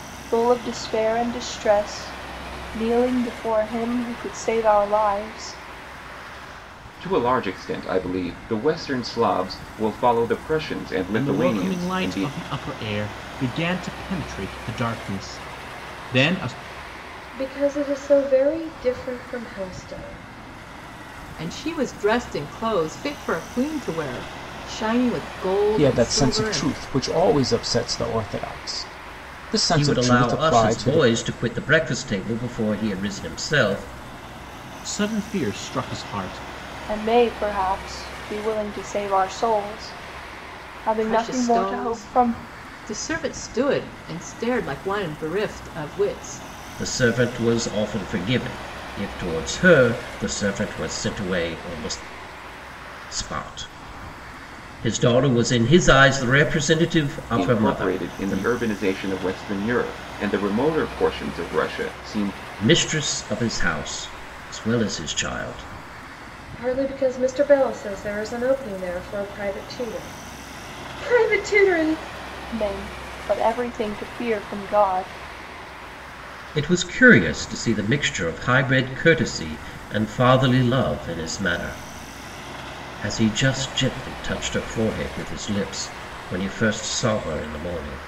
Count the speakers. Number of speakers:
7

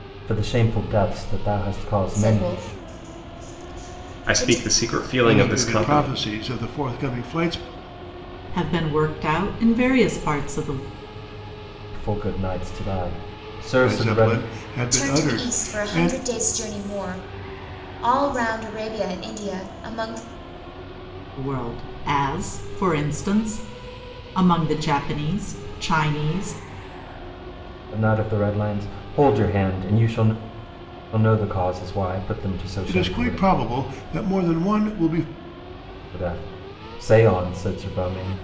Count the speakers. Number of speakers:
5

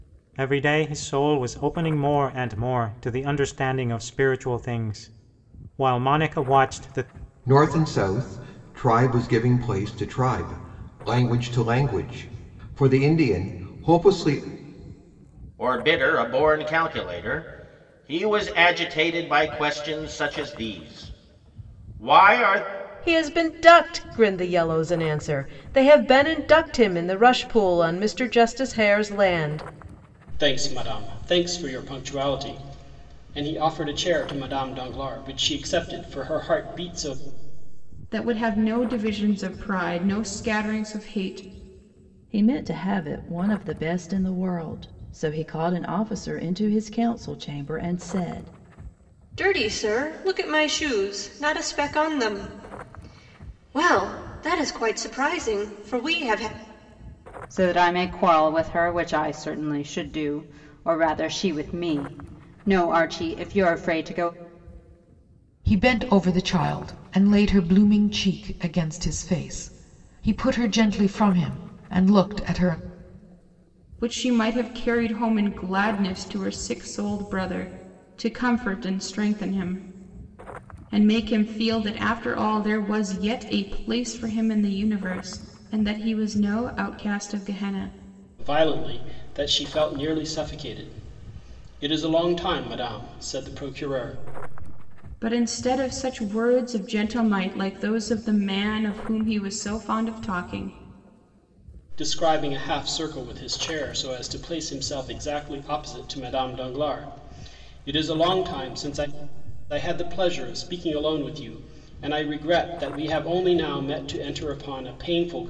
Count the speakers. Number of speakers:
10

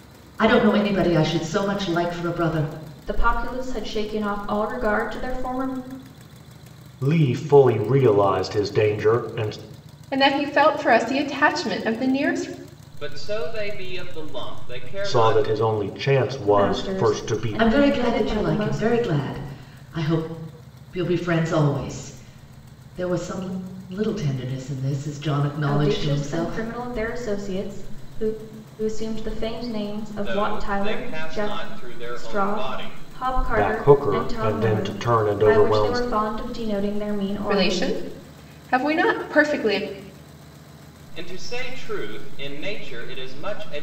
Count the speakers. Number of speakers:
5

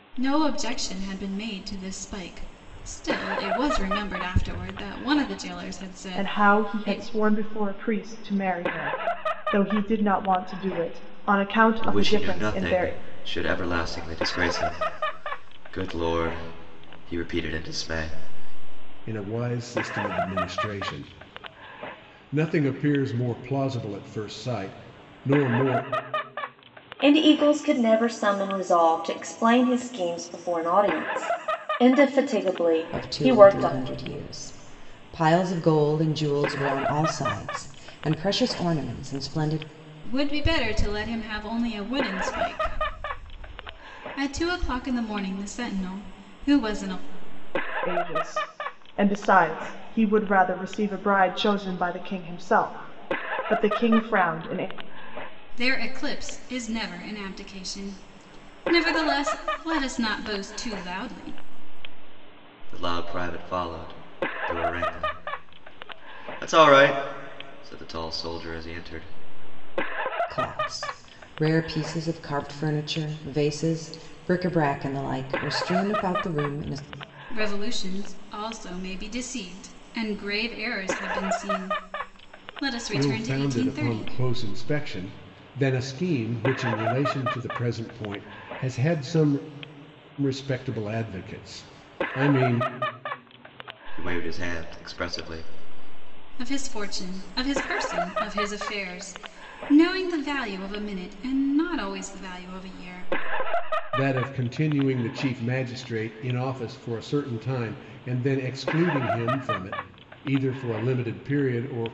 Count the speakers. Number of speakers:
6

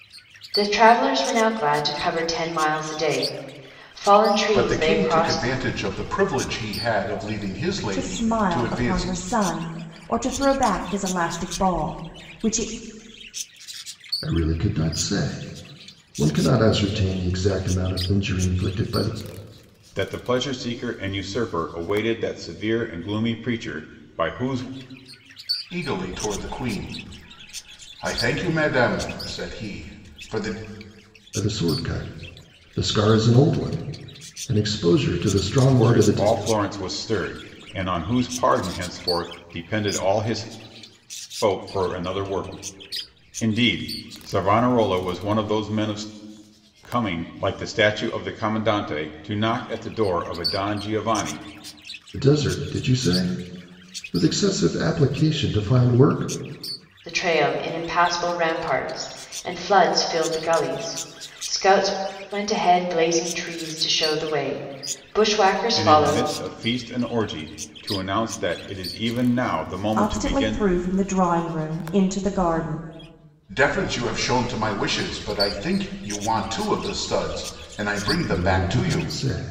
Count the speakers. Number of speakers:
5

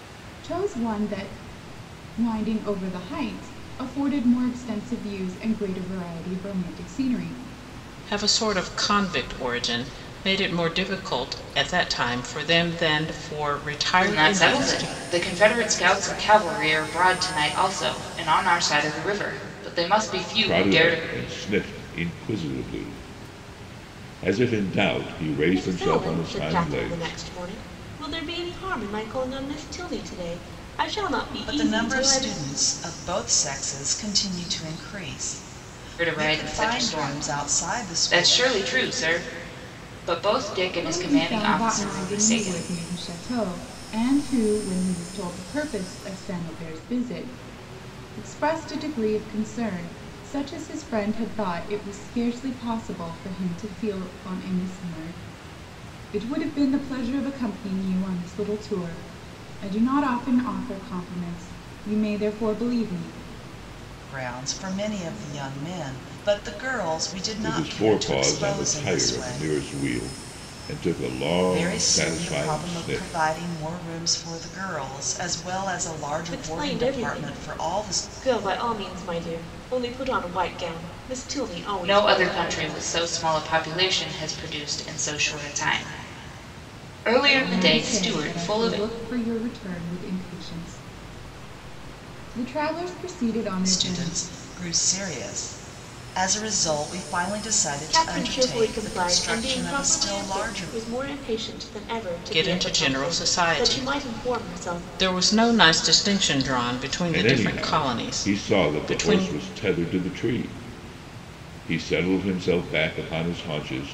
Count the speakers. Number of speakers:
6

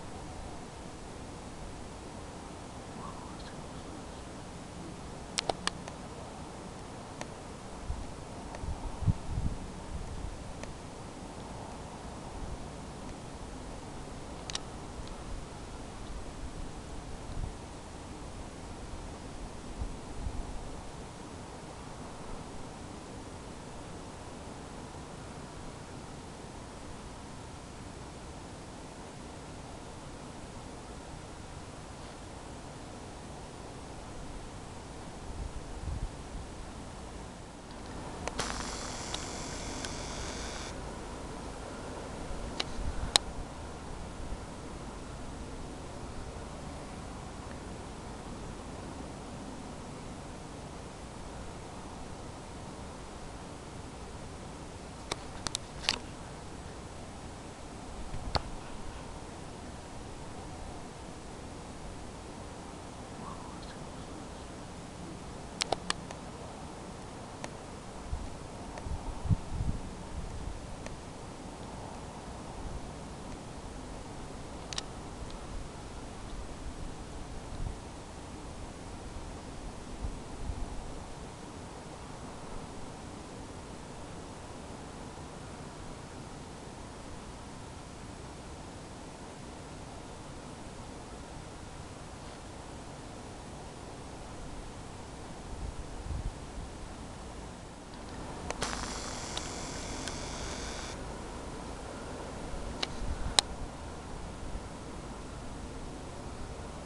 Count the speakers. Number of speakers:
0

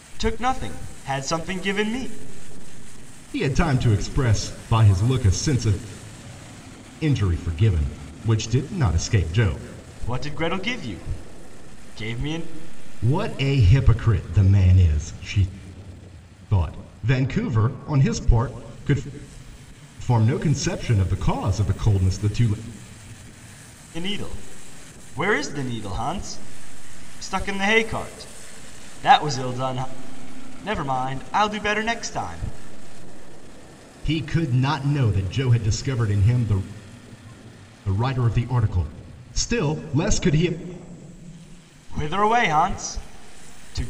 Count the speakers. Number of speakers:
2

